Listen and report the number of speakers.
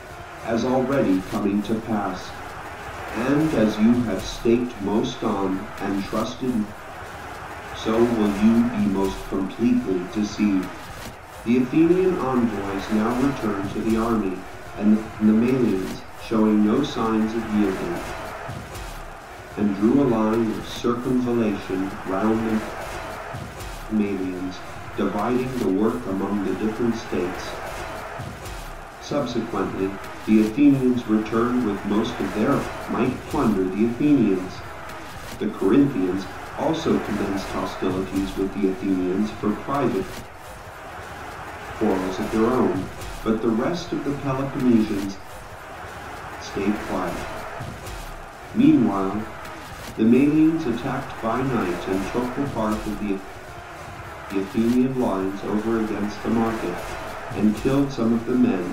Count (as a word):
one